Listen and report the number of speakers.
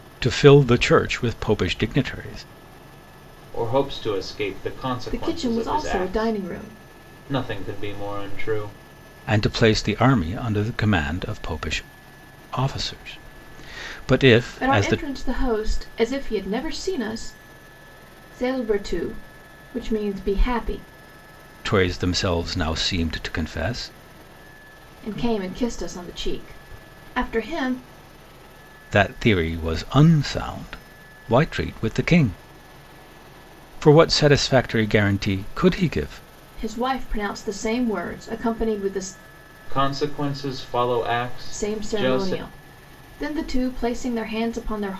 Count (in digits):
3